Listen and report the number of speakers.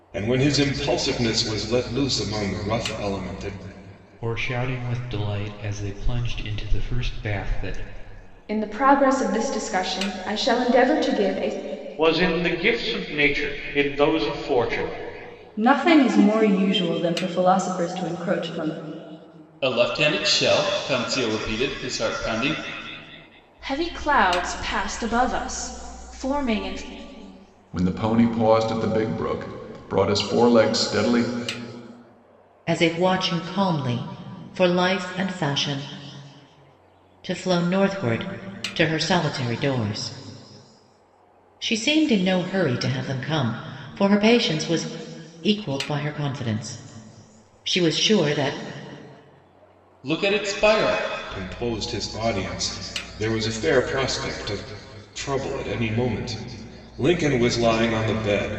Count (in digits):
9